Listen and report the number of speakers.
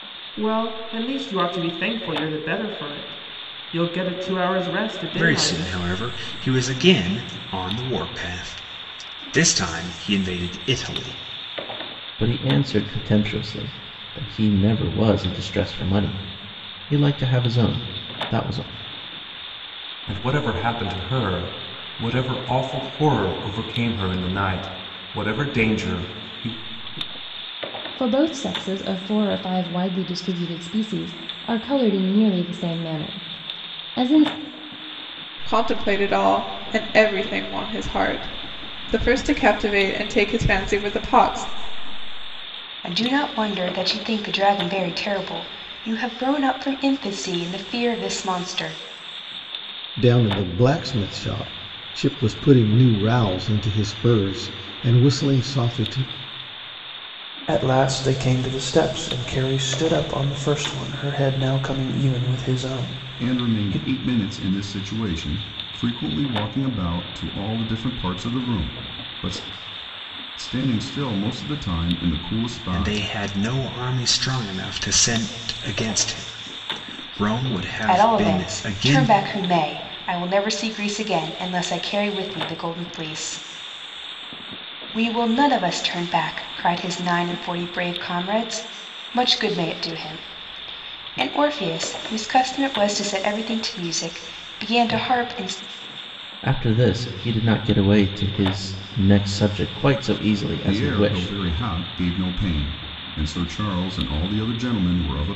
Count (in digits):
10